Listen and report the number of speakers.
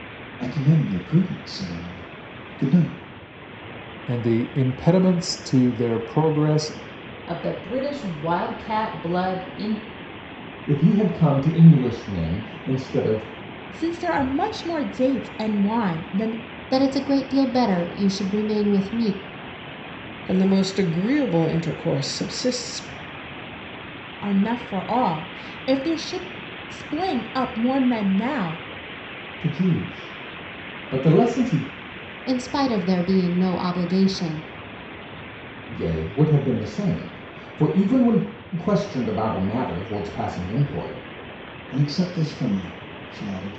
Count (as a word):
seven